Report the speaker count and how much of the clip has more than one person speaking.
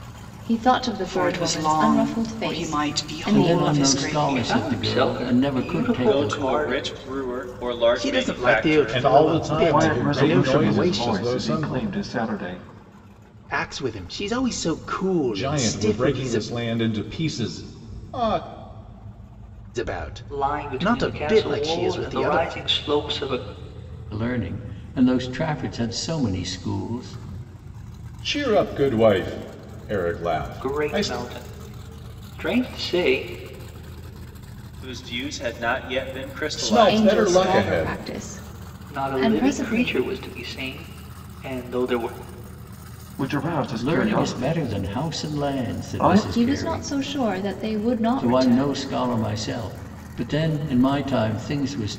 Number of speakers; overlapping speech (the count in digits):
8, about 38%